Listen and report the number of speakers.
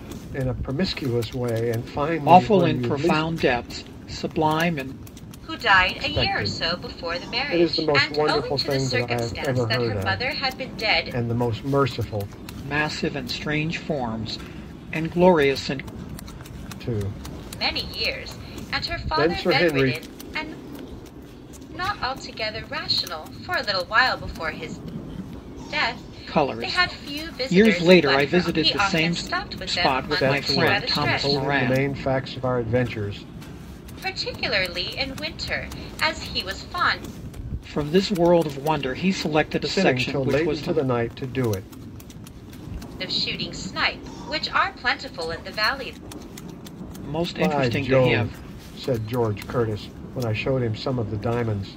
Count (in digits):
3